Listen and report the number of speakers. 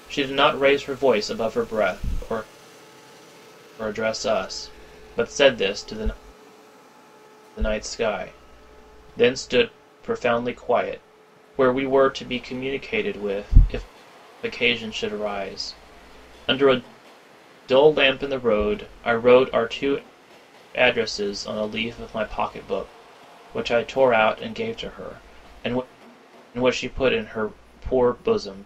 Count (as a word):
one